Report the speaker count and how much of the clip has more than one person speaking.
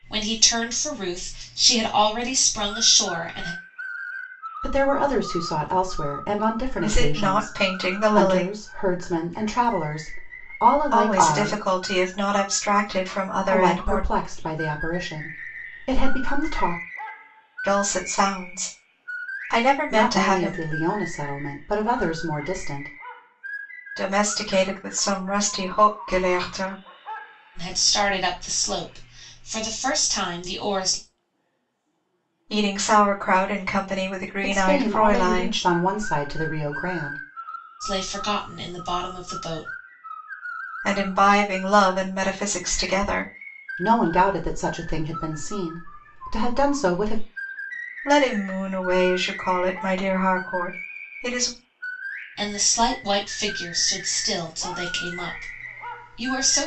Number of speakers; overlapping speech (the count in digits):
3, about 8%